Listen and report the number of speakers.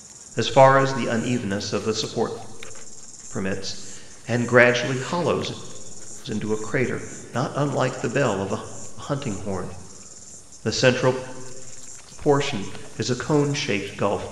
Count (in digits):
1